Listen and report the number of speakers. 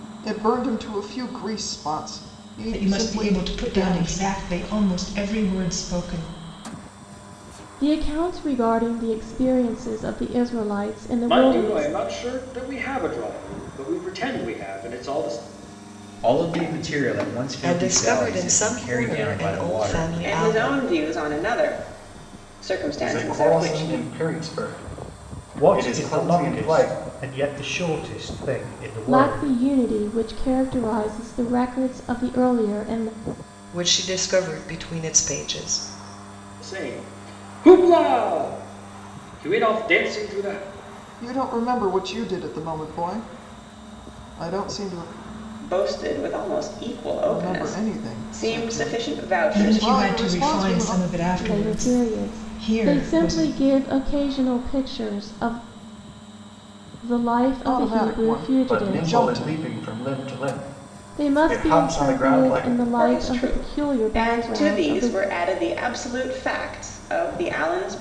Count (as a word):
nine